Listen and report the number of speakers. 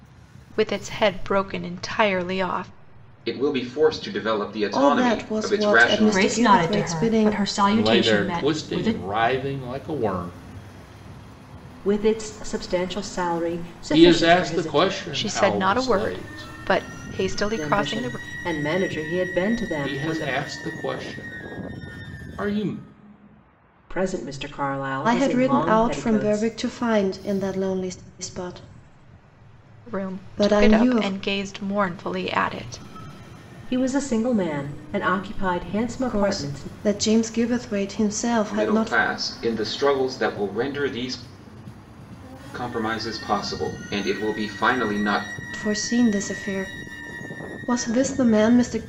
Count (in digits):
6